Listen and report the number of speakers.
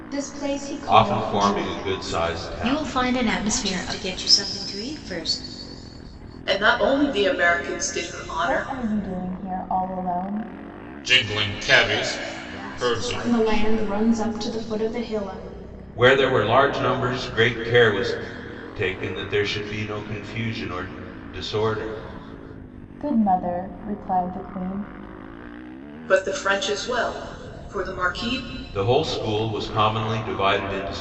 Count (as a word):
eight